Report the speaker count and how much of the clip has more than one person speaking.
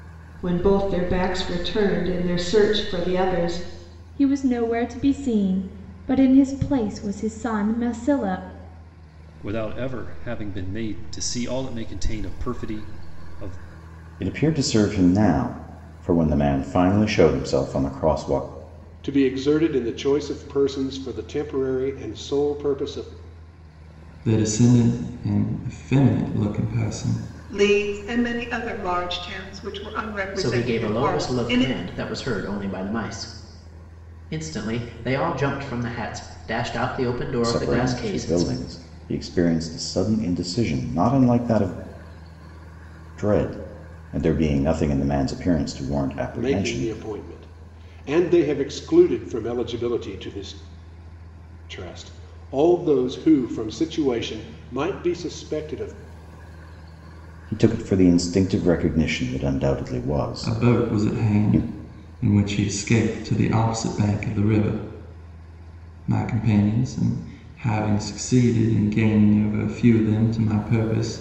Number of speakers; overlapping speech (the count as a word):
eight, about 6%